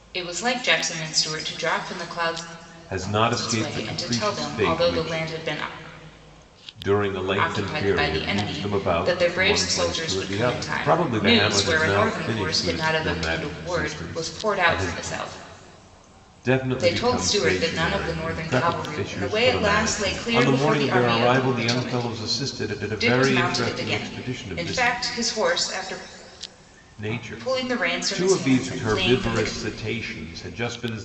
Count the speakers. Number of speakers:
two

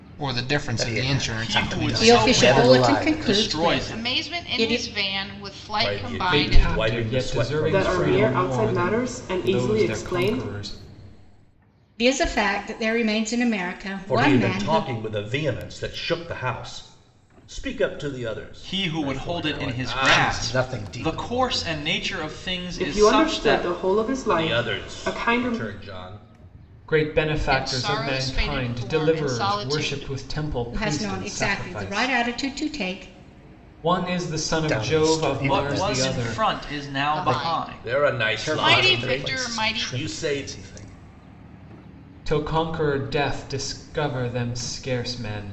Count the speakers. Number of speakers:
eight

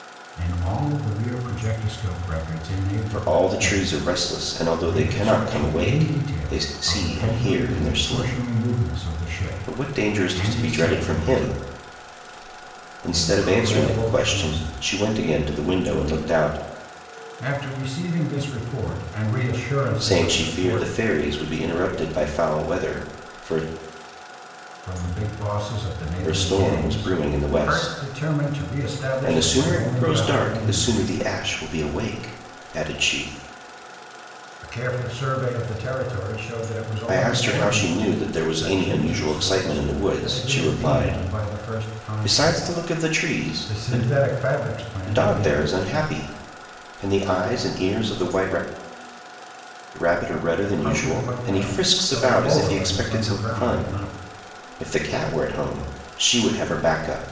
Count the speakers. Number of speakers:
two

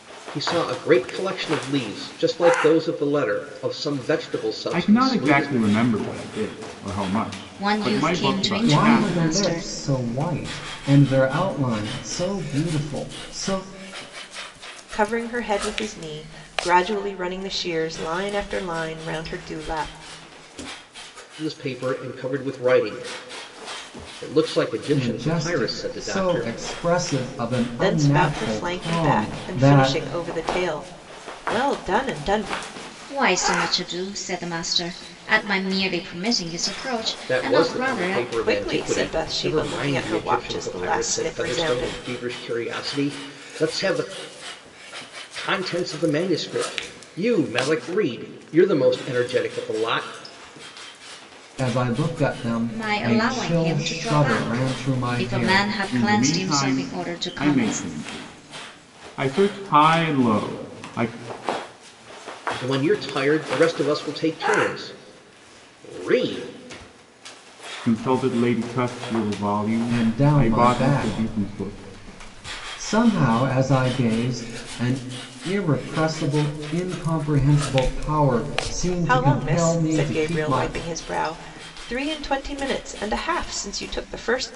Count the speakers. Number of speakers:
five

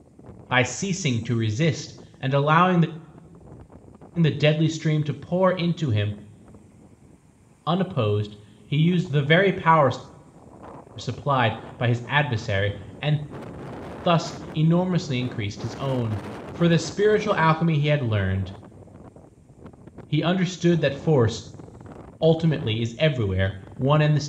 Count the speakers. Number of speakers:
one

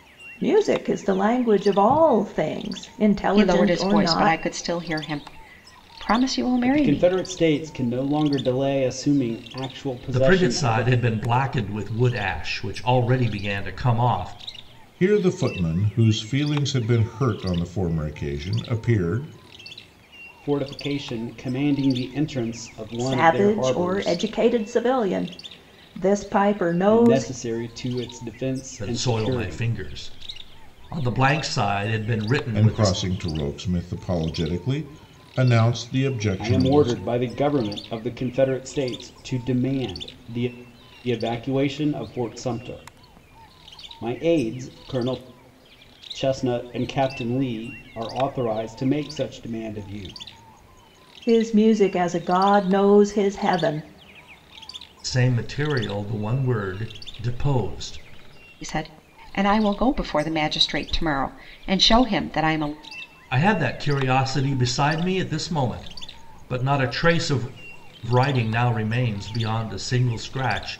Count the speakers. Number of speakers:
five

